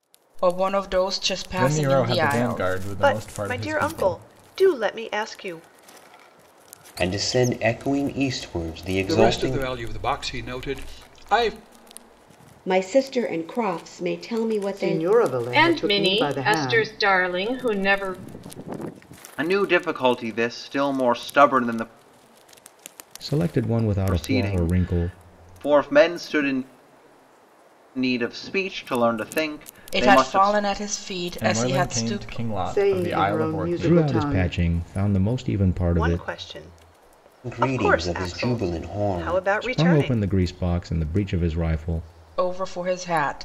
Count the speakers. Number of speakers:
ten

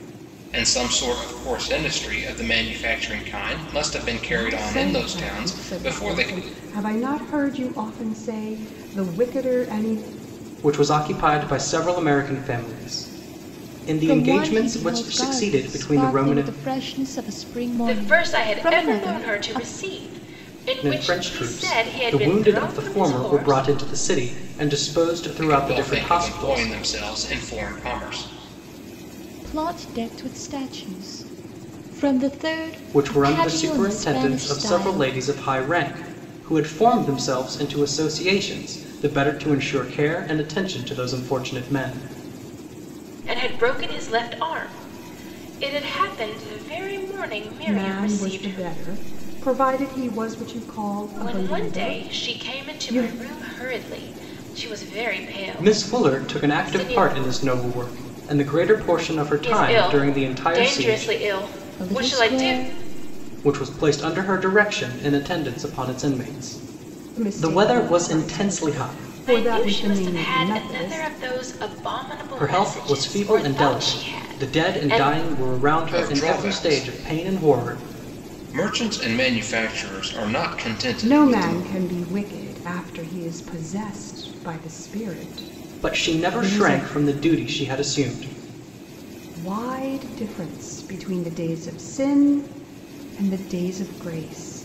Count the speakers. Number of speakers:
five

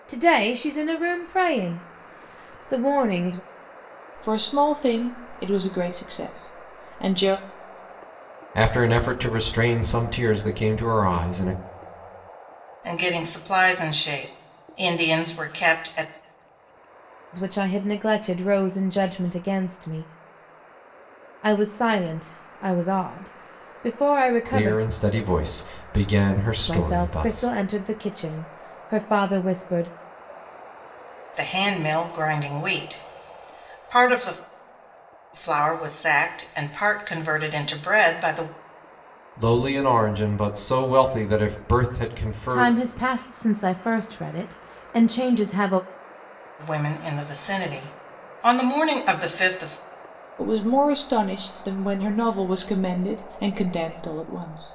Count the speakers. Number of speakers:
four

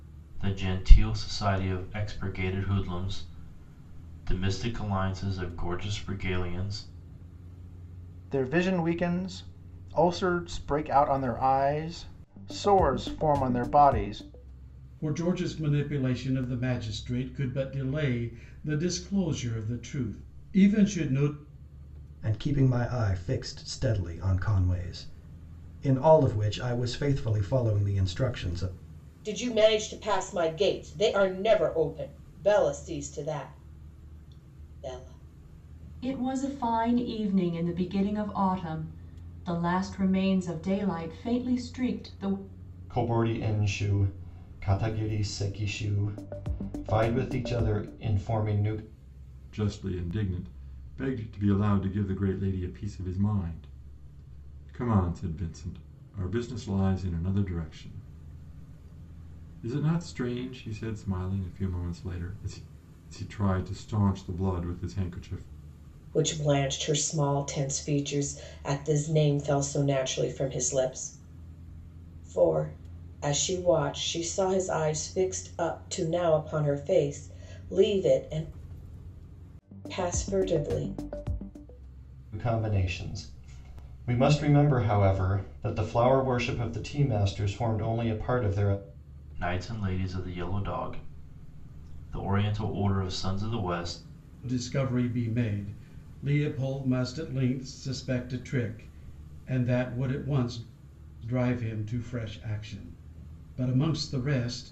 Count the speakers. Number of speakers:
eight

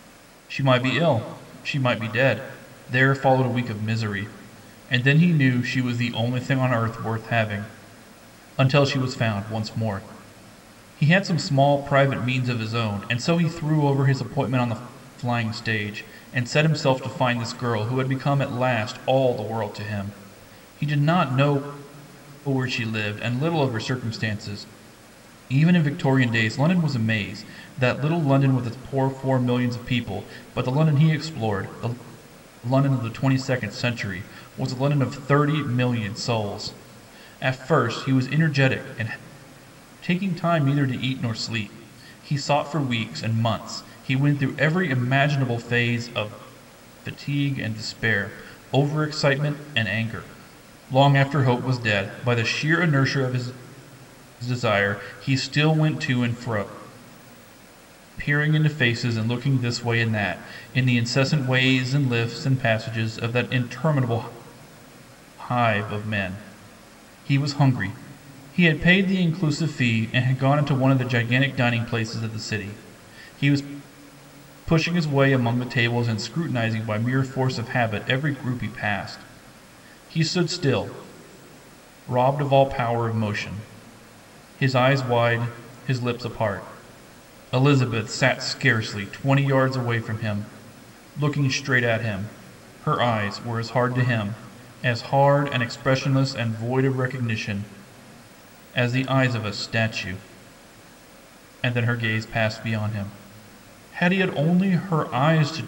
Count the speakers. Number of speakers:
one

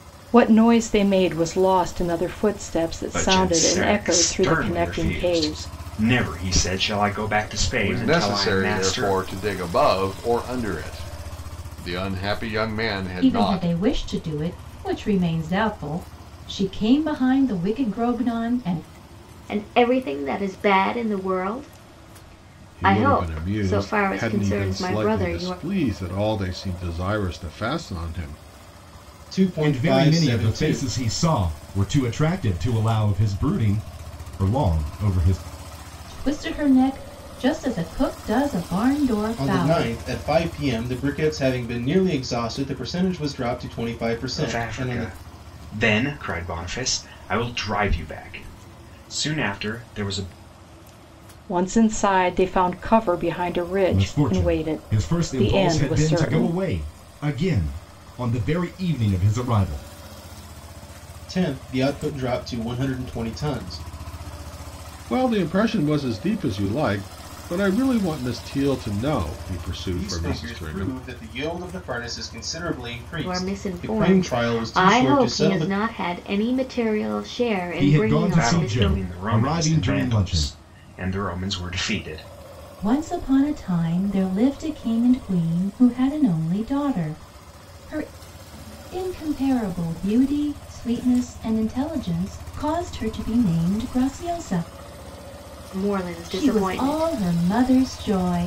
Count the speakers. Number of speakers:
eight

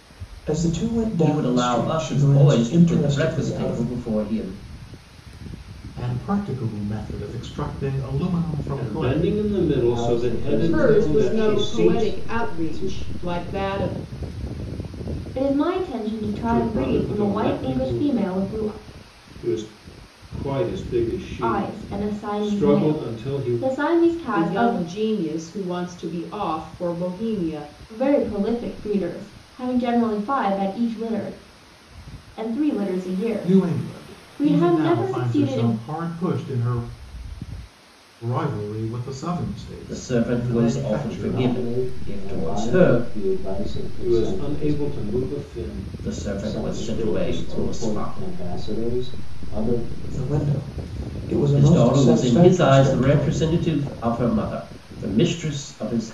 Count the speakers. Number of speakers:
seven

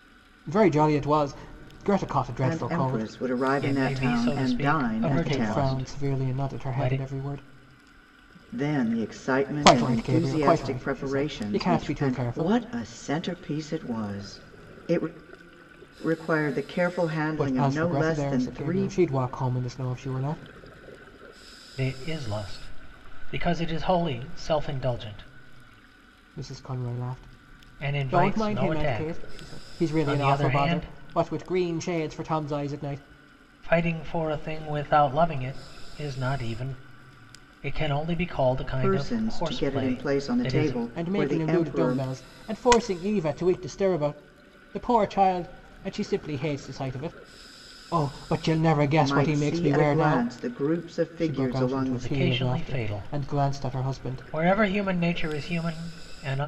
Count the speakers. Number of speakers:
three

